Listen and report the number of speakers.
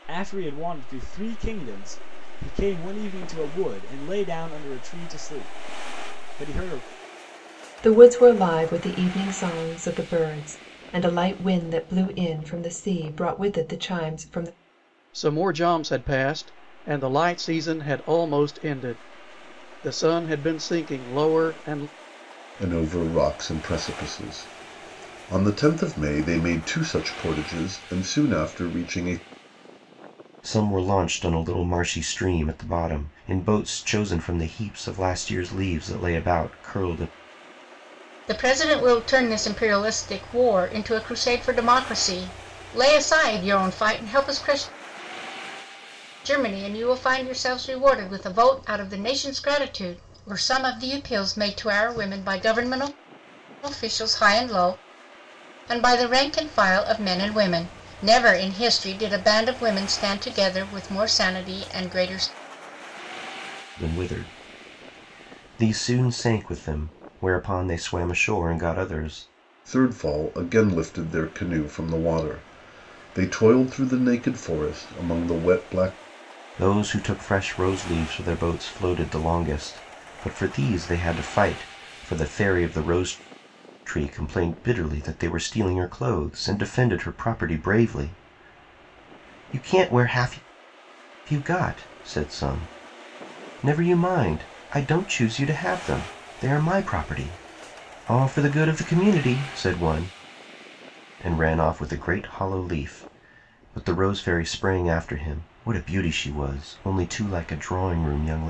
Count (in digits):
6